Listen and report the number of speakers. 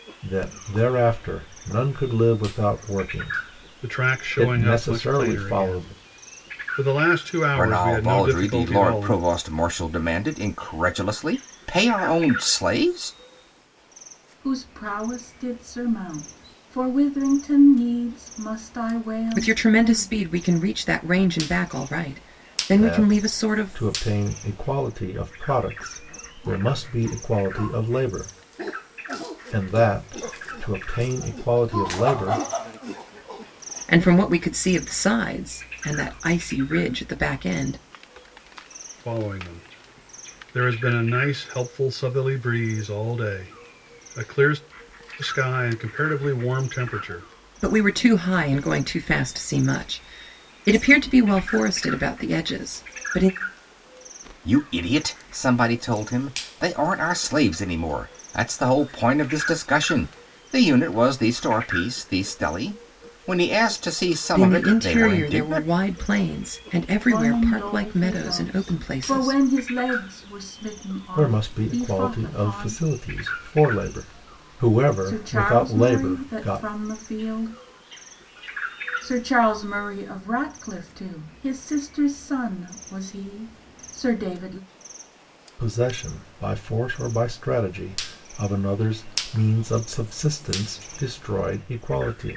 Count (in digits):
5